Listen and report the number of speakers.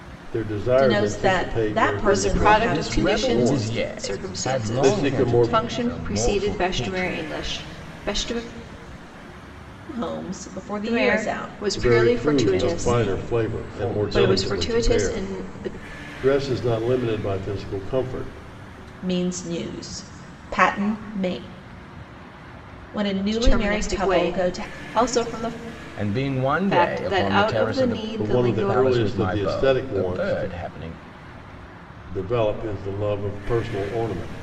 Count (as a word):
four